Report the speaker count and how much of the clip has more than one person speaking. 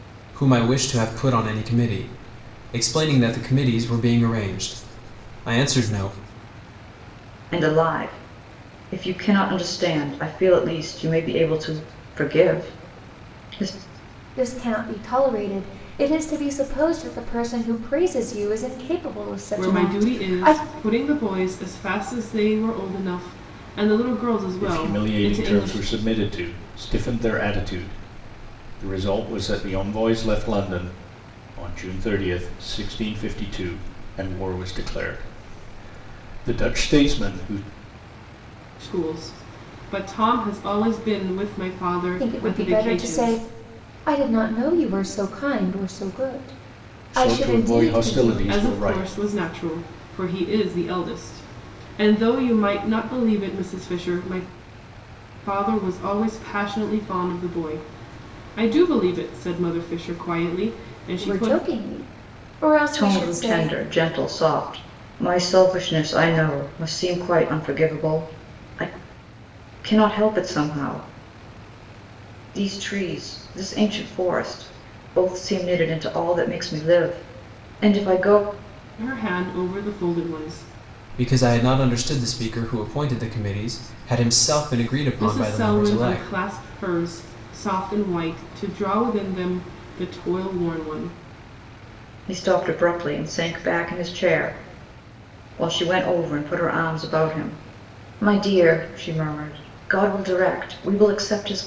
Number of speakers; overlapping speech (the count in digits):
5, about 8%